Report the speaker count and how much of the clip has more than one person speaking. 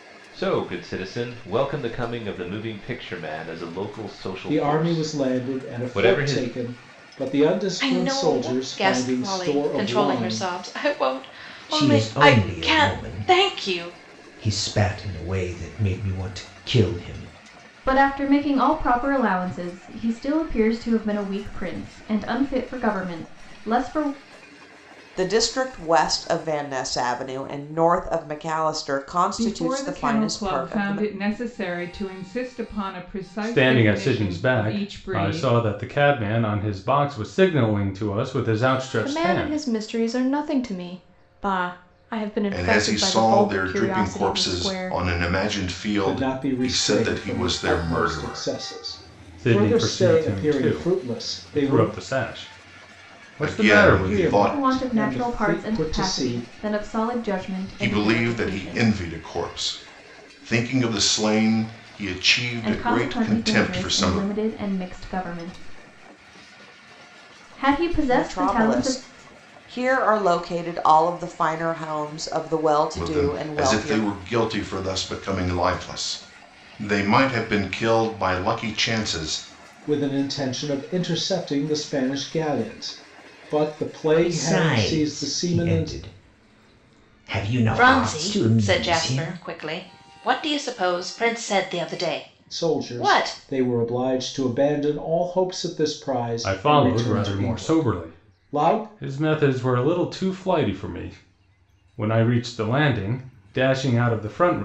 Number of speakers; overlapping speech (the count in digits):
10, about 32%